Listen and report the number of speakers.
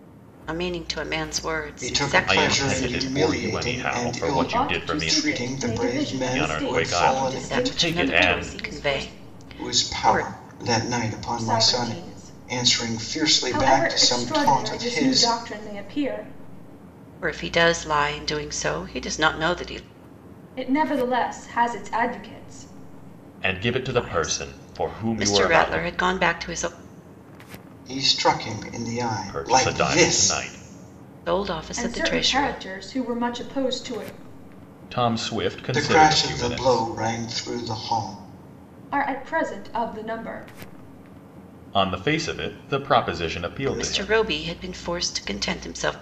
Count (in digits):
4